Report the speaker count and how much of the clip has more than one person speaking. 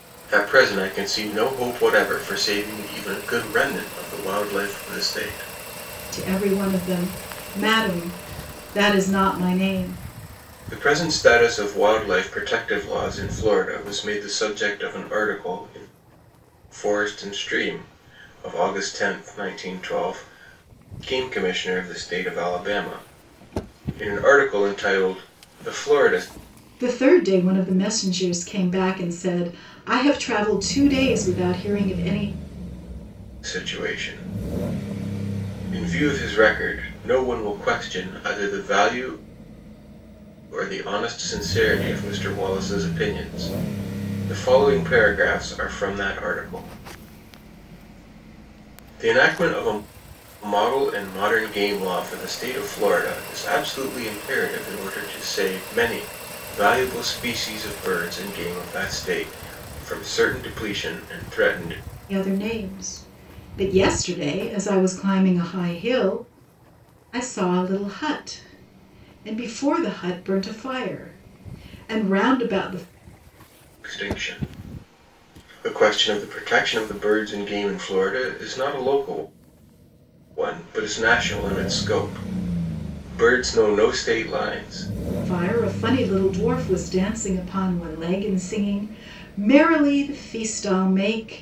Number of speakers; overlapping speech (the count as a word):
two, no overlap